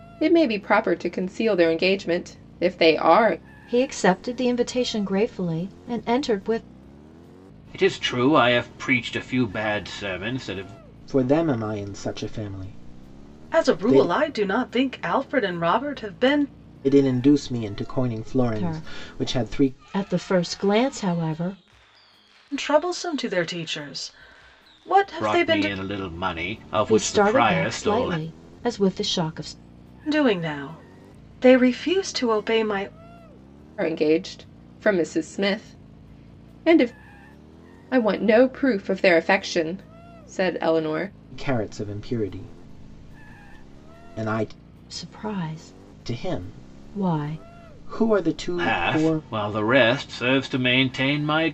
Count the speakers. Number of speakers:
five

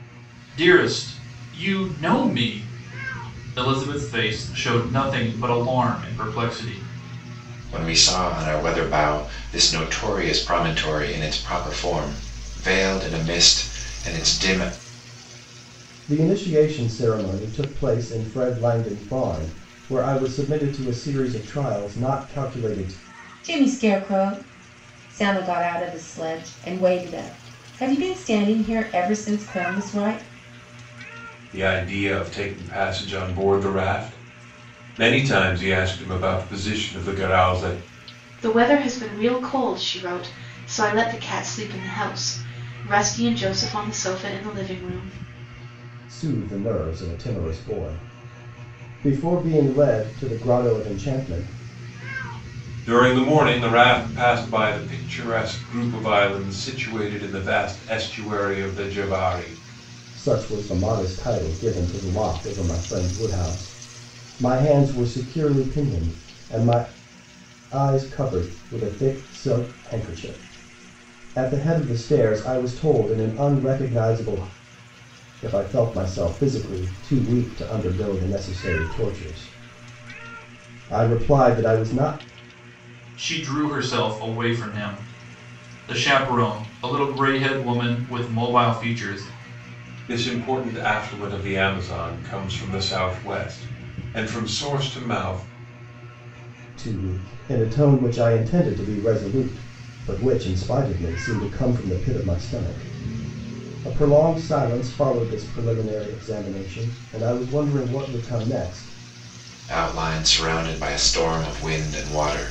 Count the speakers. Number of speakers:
six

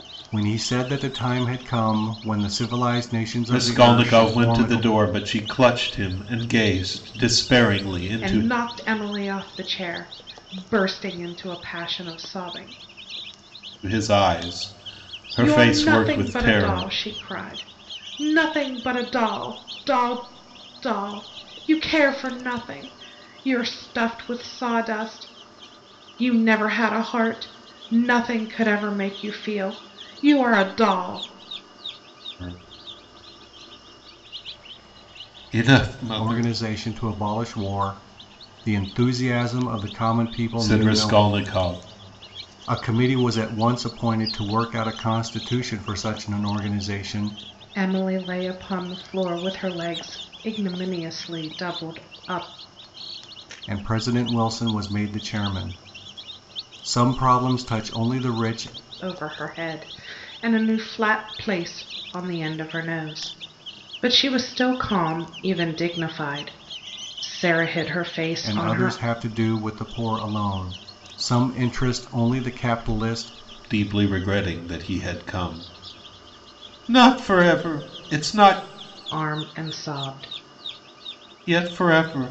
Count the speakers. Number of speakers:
three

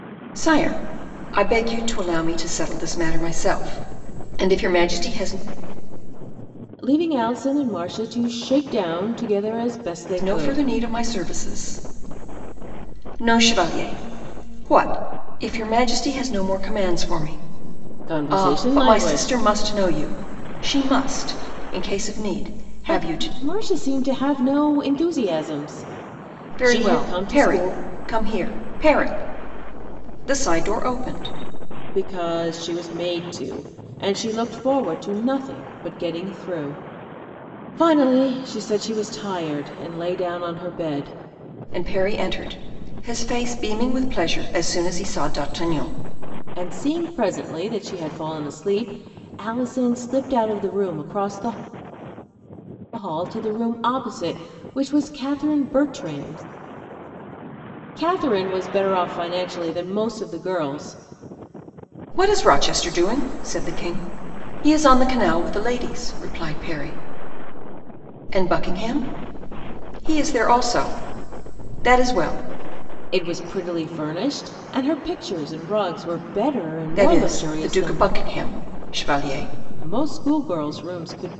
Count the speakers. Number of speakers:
two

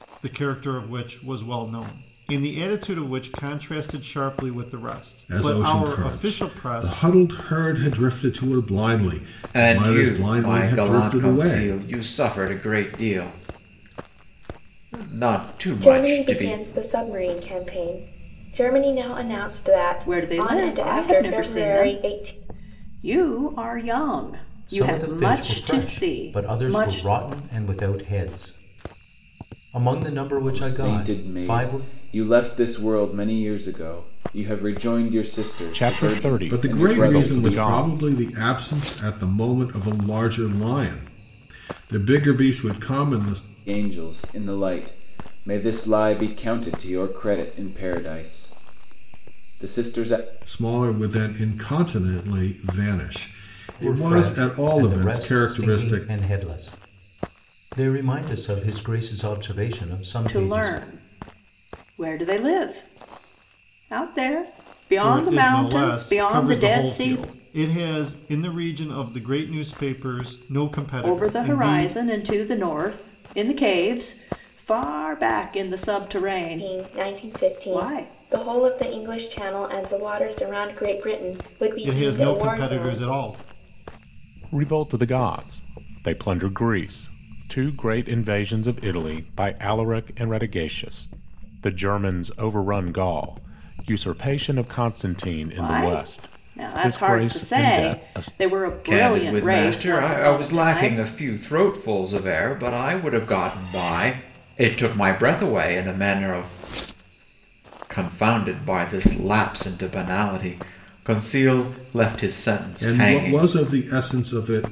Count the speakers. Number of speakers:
eight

